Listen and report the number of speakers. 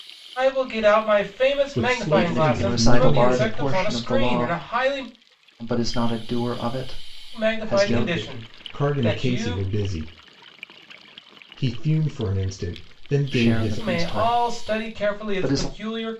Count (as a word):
three